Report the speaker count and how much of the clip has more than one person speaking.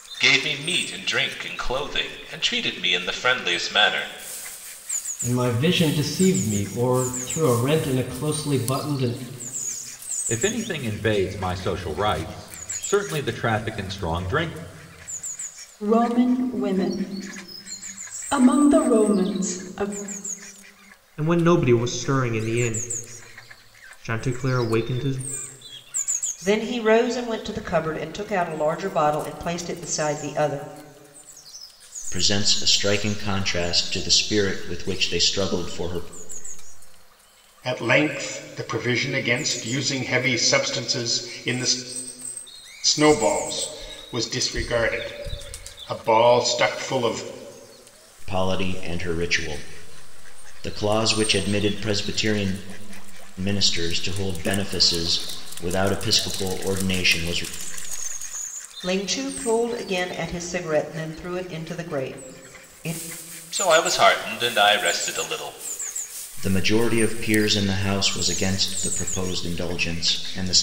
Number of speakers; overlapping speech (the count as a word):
eight, no overlap